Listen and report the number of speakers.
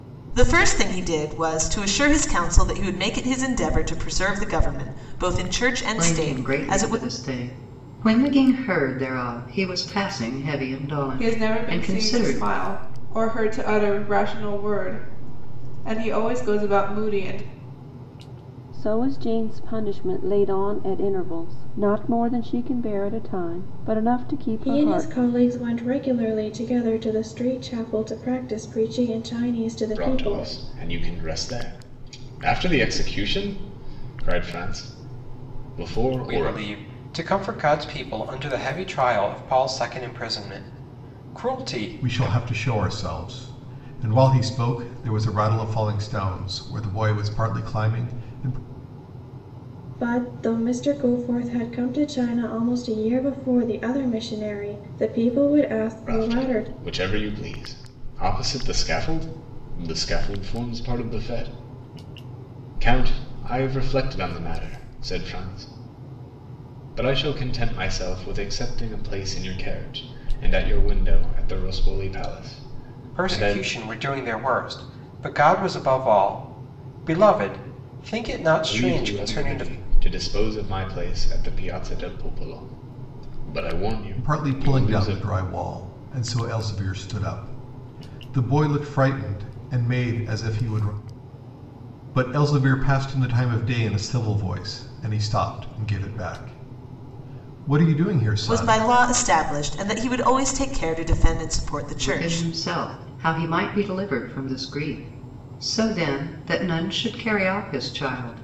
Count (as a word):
eight